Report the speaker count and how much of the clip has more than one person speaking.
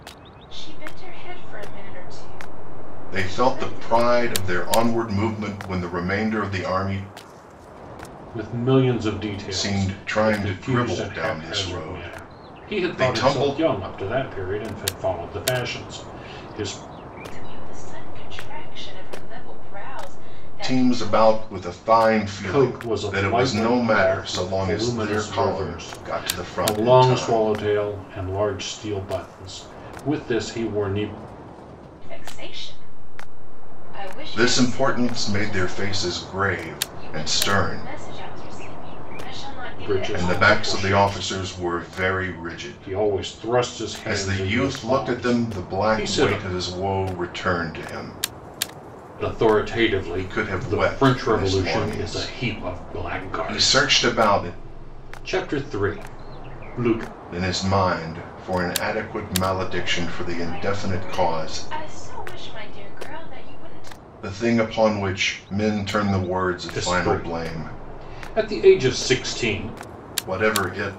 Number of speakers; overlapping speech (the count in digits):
3, about 38%